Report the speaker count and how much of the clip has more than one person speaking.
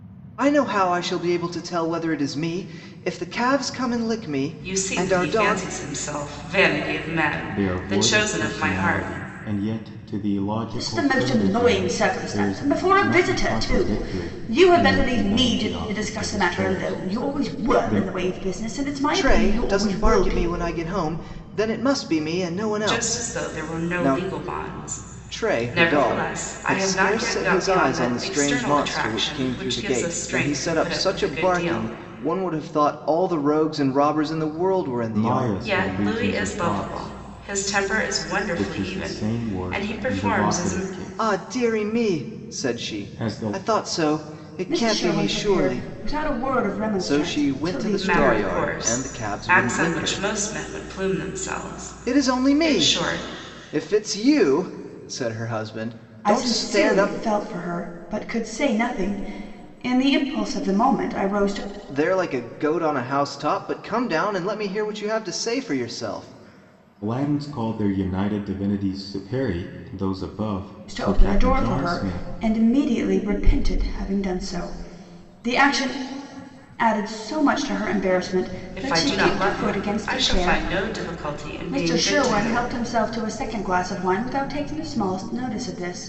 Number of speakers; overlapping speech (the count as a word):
four, about 43%